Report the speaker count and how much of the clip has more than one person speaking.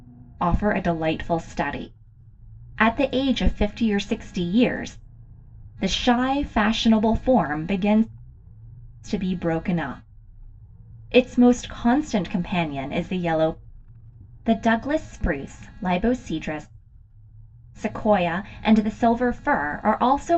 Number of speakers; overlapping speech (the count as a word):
one, no overlap